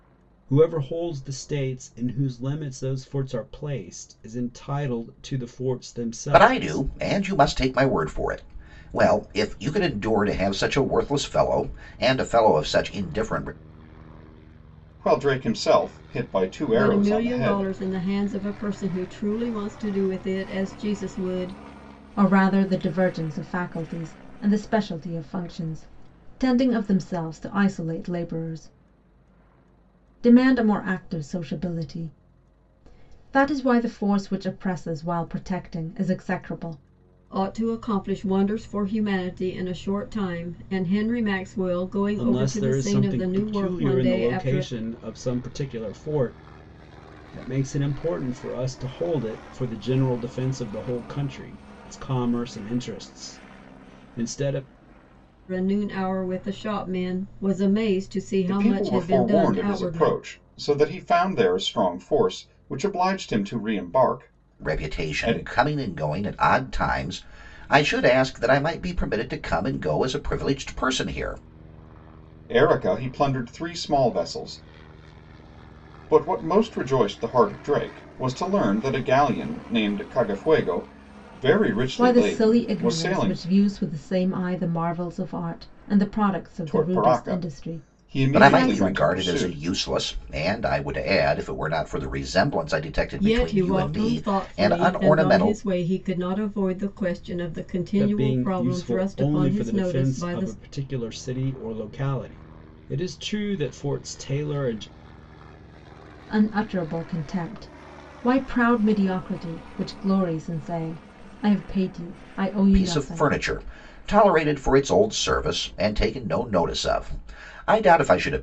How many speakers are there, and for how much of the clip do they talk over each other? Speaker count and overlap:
five, about 14%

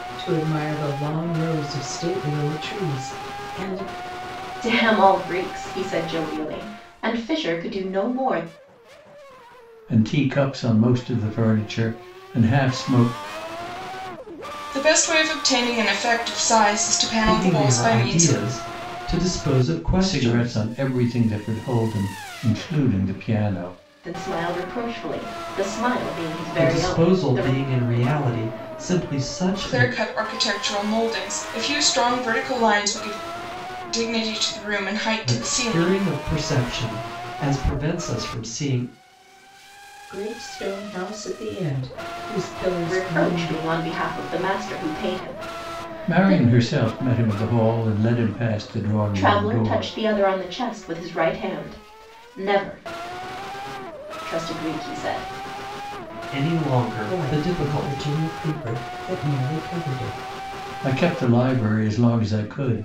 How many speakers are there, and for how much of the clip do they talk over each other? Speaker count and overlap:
five, about 11%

